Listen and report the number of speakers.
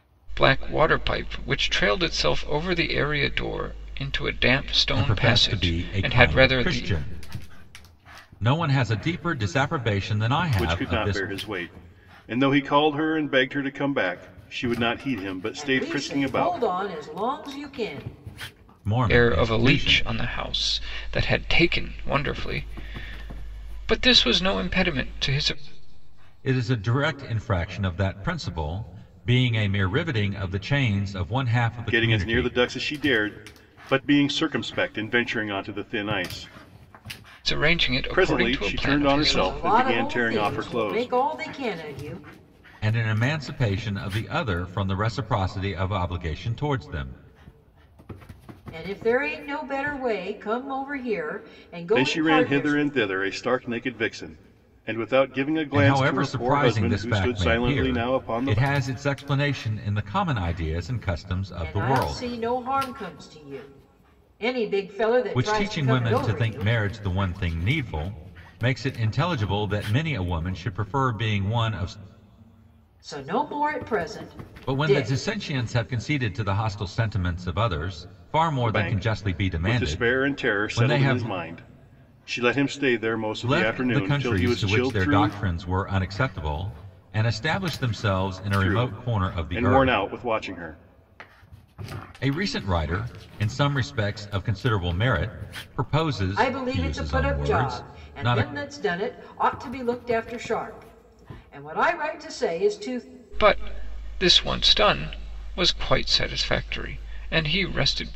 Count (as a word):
four